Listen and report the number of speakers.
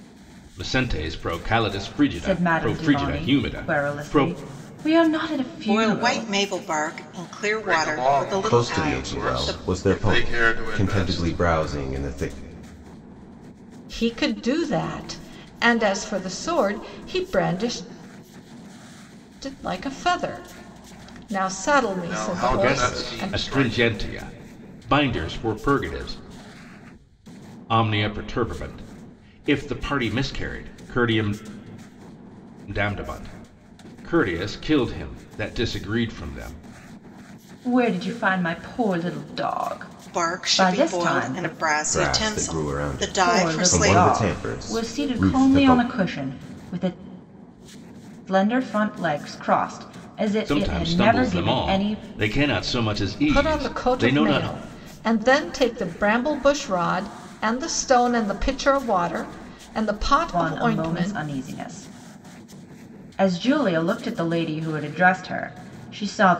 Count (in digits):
6